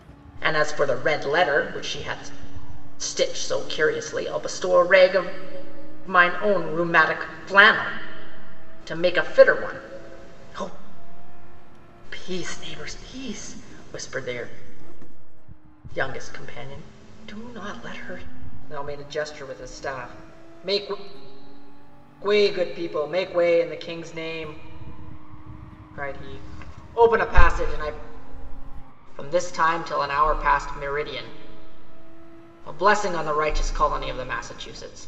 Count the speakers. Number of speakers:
one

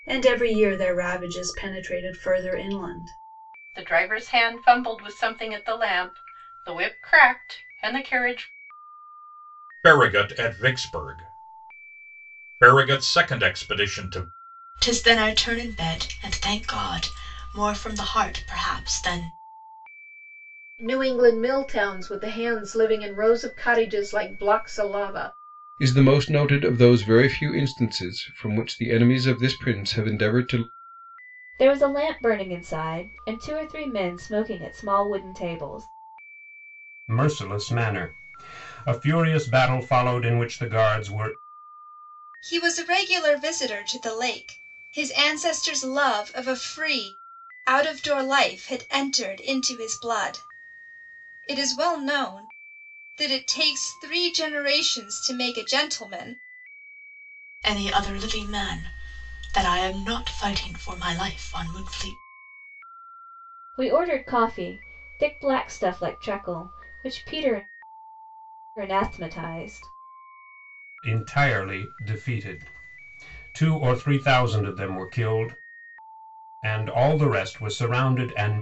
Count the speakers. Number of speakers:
nine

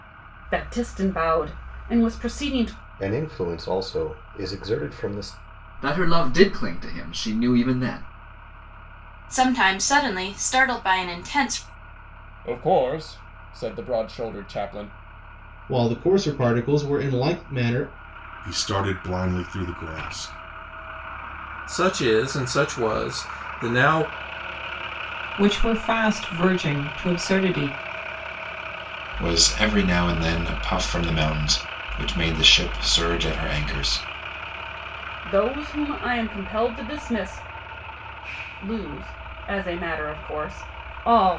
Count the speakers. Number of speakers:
ten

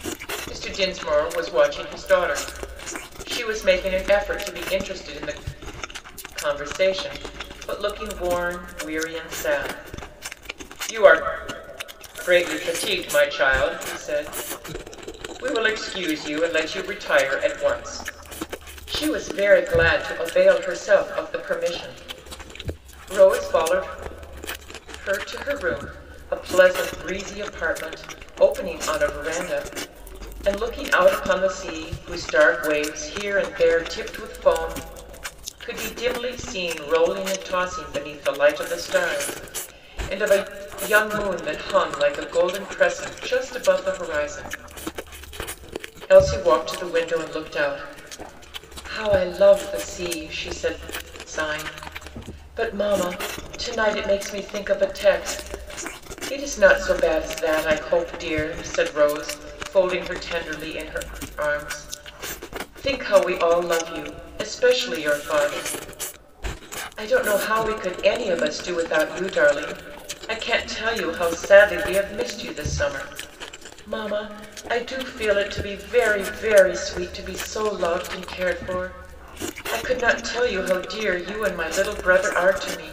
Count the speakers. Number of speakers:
one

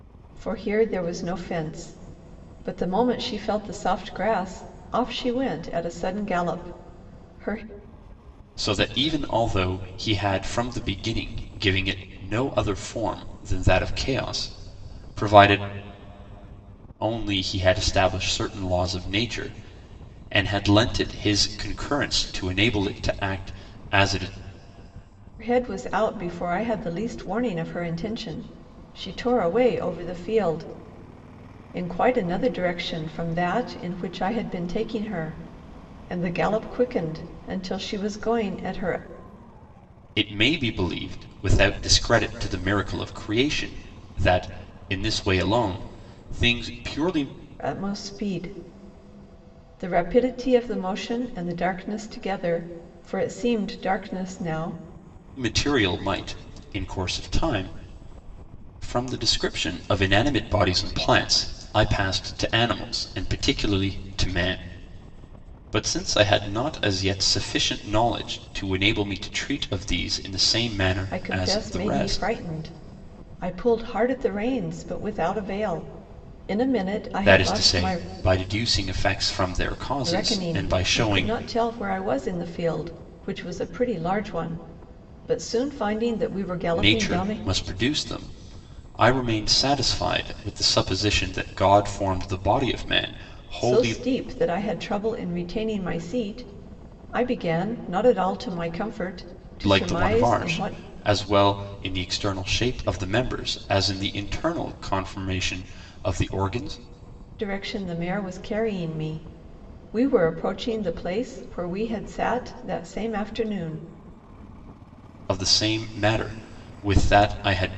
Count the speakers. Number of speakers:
two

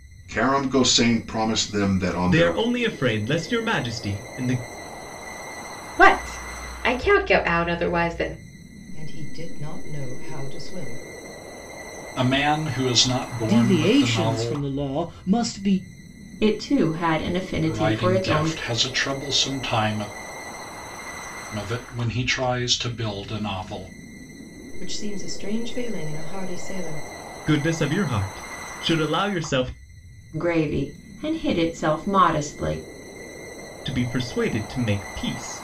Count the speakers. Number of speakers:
seven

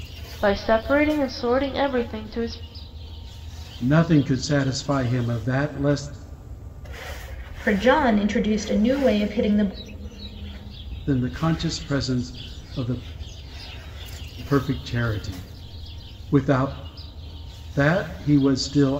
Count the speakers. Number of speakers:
three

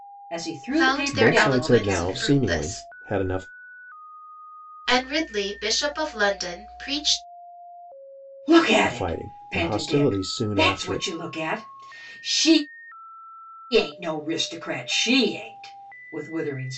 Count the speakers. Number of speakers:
three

